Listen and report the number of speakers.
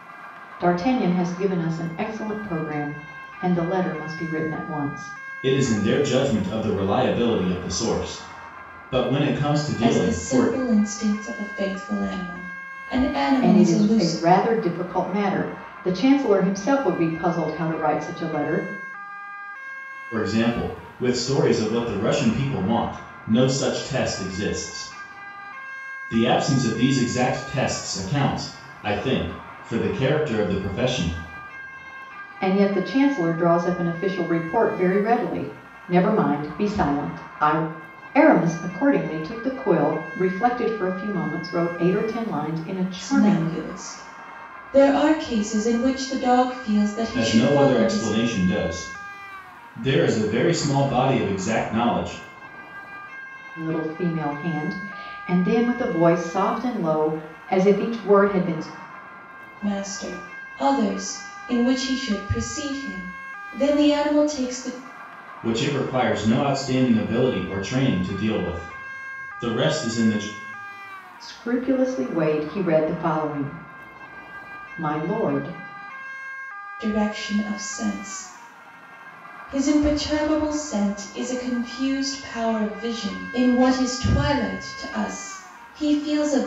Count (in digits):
3